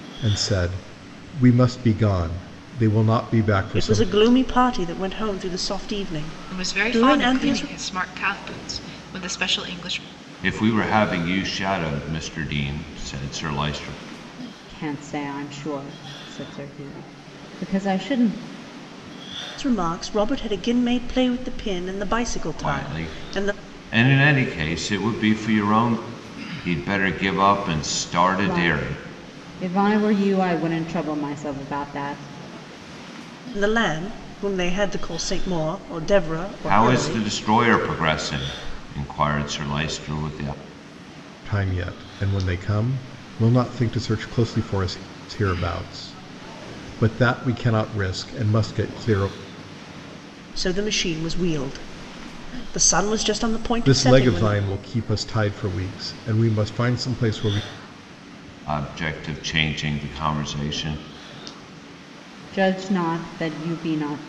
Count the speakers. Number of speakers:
5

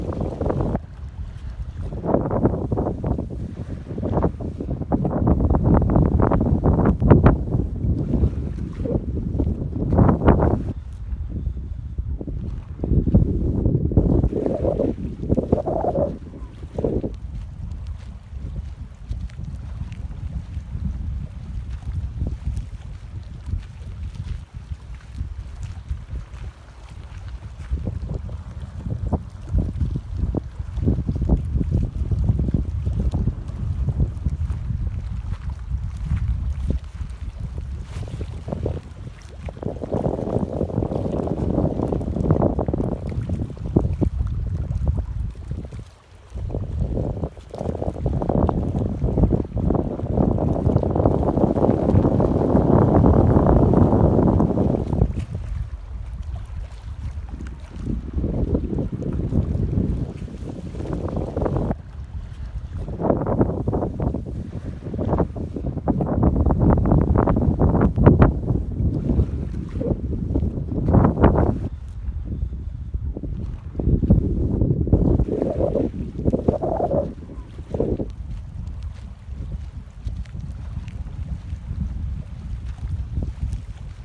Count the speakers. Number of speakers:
0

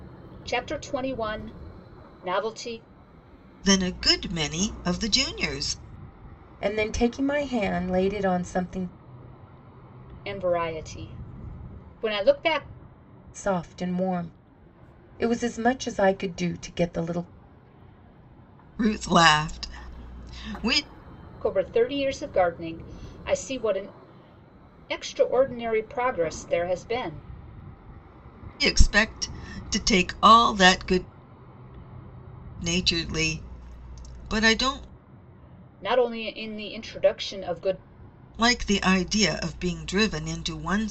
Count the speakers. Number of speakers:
3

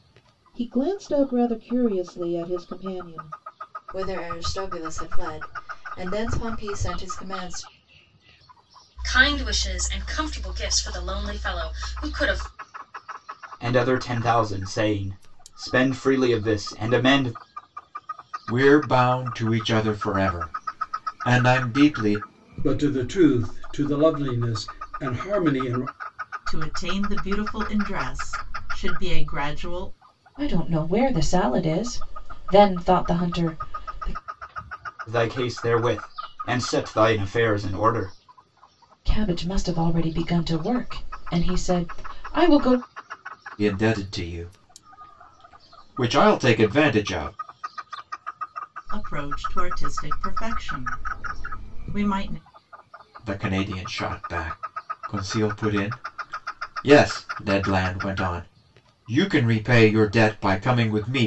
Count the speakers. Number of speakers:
8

